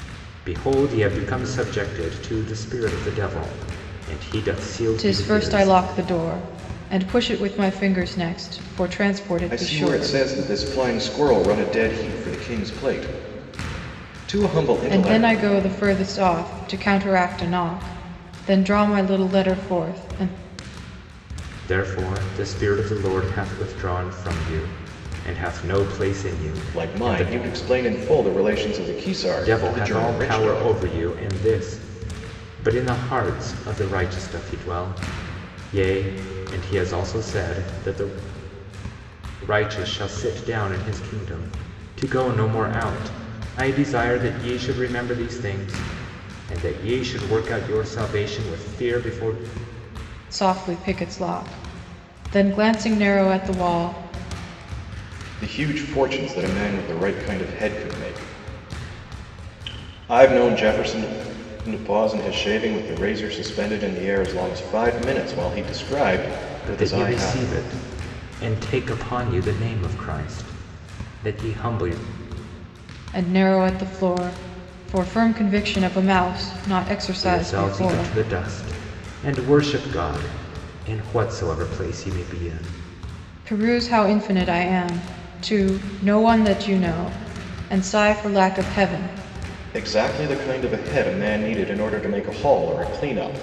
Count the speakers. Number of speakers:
three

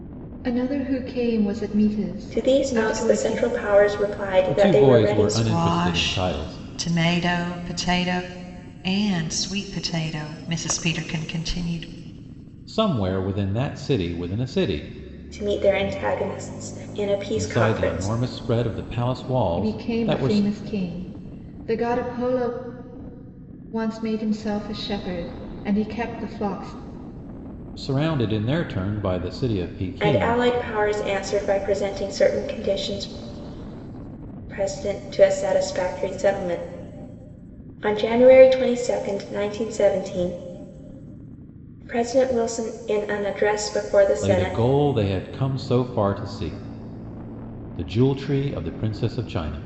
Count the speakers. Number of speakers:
four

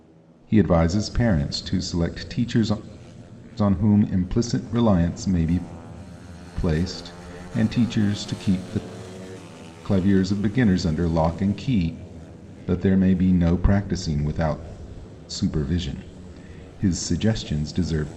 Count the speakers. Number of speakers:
one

